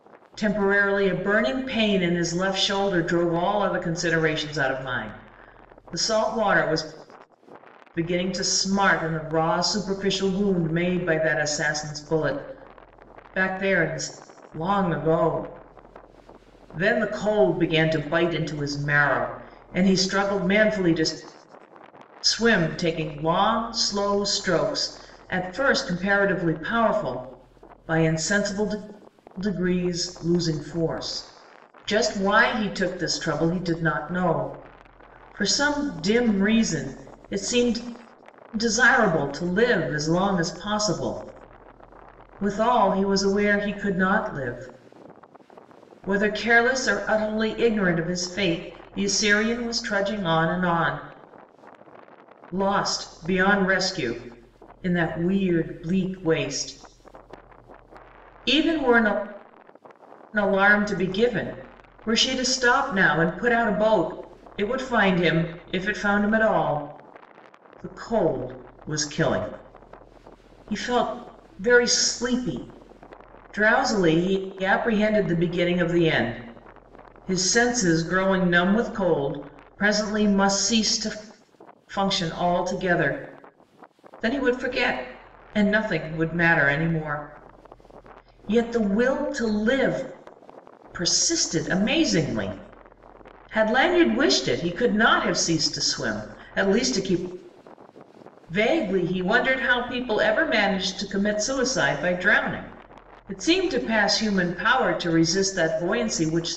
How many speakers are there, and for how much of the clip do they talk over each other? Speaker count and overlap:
one, no overlap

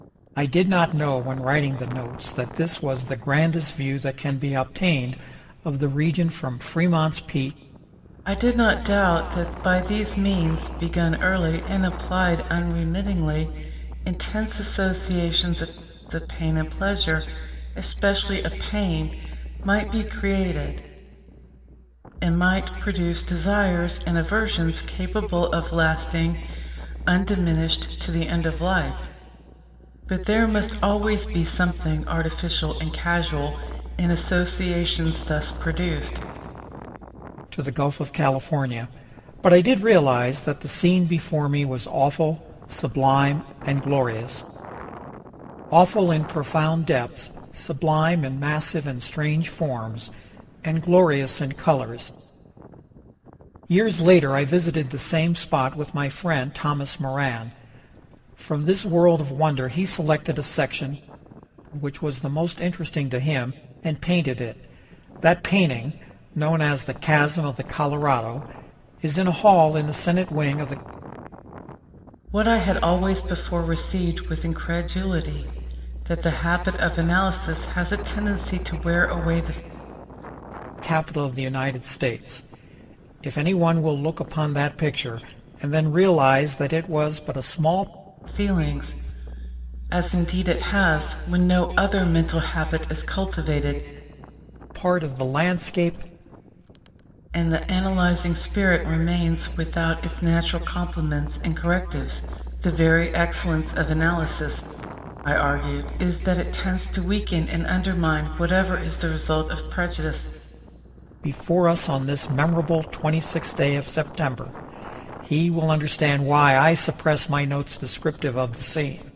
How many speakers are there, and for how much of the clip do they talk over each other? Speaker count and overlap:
two, no overlap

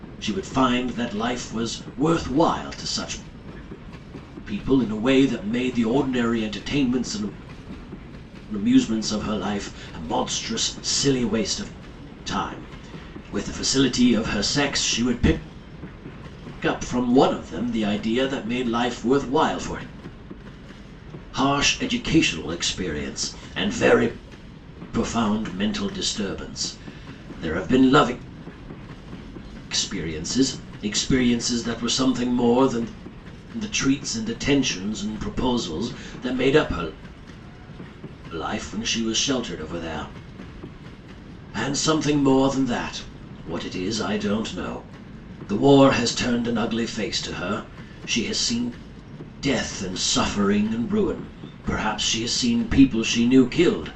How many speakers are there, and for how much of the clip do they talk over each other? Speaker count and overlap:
one, no overlap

